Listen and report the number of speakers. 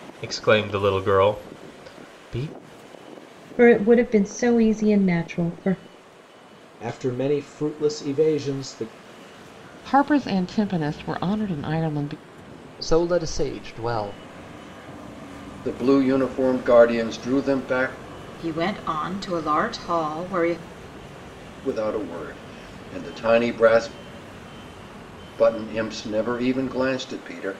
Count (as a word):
seven